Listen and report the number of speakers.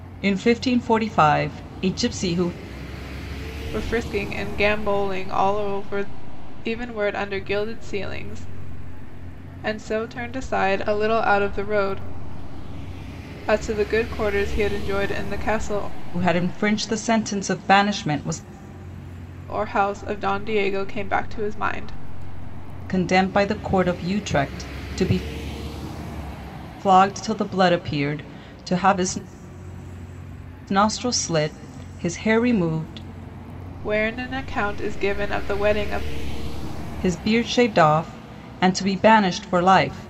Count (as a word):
two